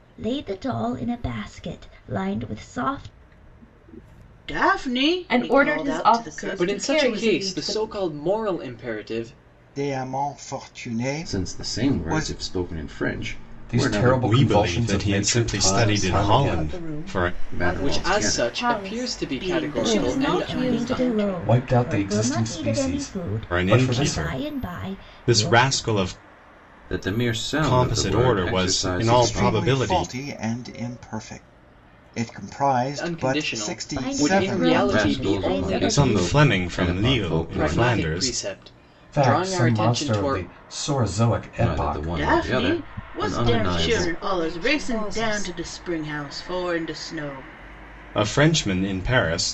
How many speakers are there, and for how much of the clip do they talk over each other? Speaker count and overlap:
9, about 58%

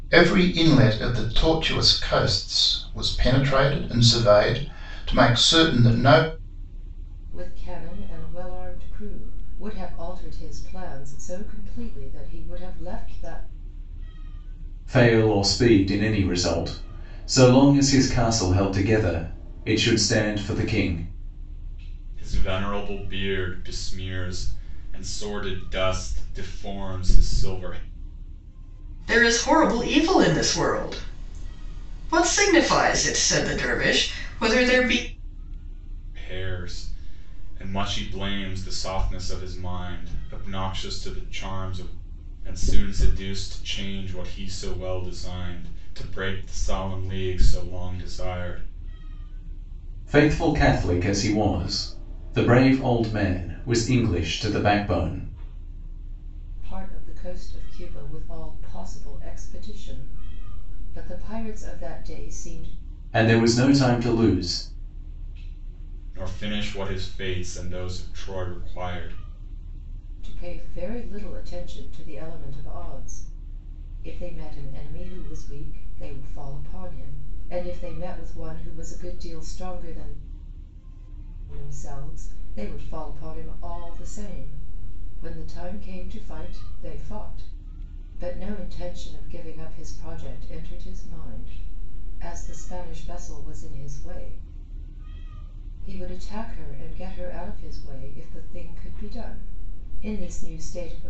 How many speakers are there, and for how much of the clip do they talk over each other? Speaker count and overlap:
5, no overlap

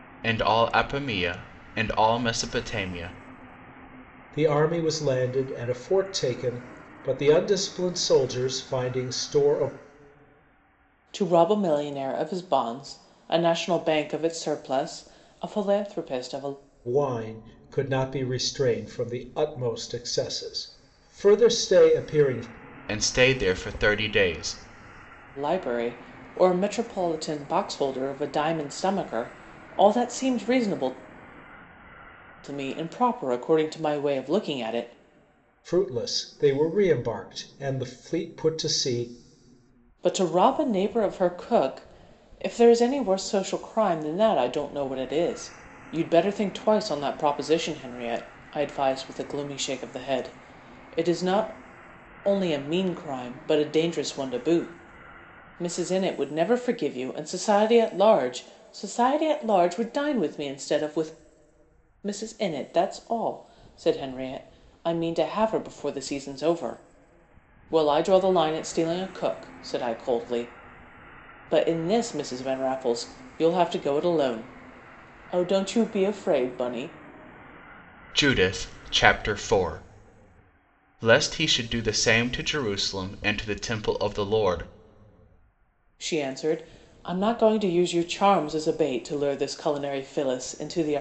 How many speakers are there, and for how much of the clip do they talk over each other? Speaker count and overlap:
3, no overlap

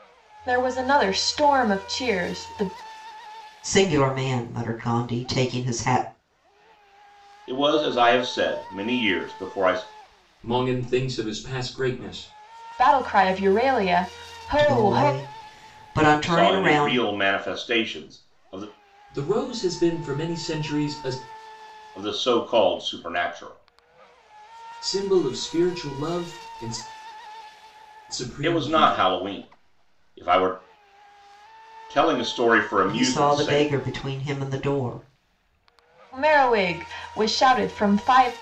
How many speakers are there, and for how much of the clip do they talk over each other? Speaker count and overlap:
4, about 8%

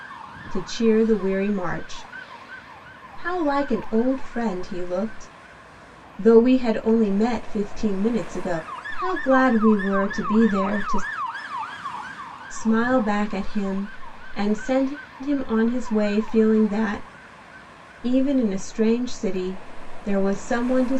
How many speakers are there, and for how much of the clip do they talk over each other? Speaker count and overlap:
1, no overlap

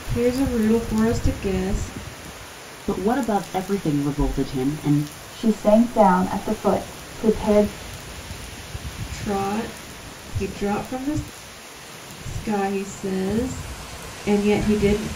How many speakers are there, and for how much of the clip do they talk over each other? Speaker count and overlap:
3, no overlap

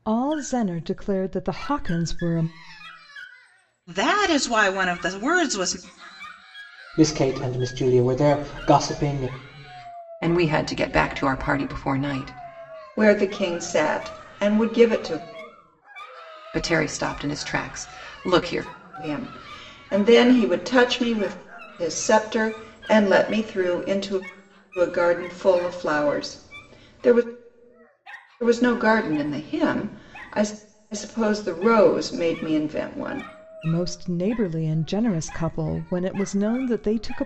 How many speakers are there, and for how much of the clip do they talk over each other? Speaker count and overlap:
5, no overlap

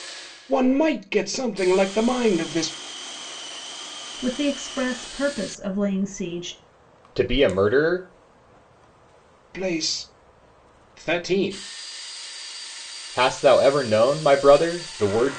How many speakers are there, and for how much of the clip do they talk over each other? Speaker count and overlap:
3, no overlap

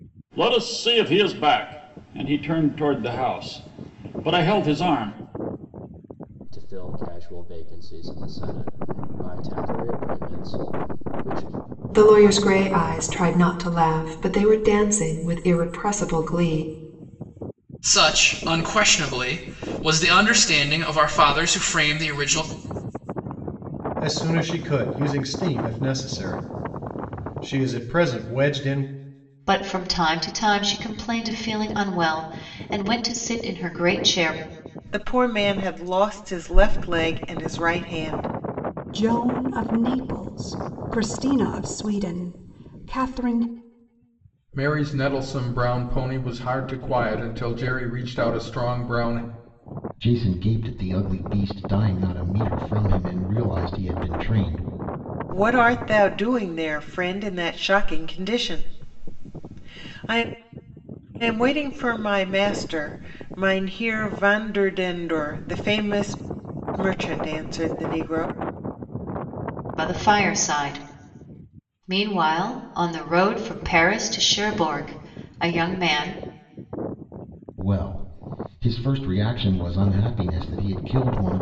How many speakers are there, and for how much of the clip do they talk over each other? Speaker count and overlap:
10, no overlap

